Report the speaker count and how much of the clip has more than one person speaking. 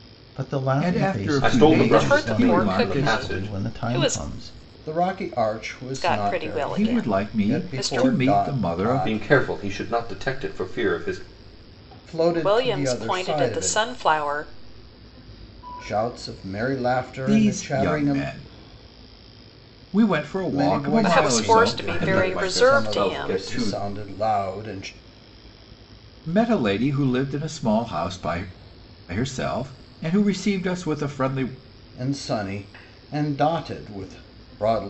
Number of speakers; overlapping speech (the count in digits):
4, about 37%